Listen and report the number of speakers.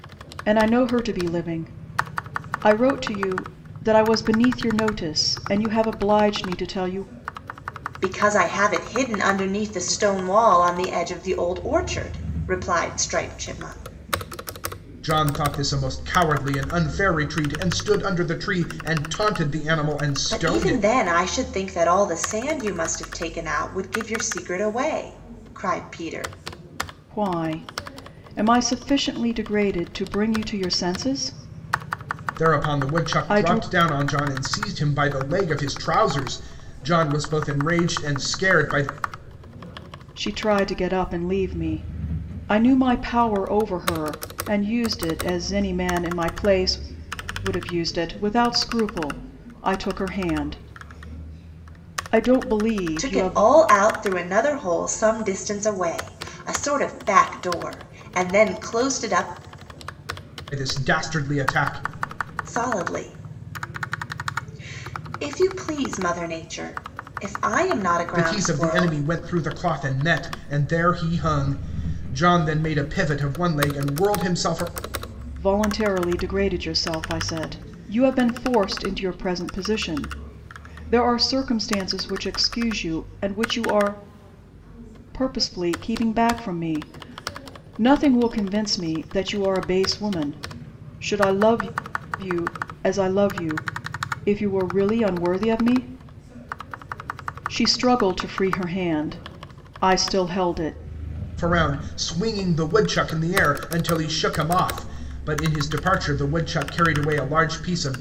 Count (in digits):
3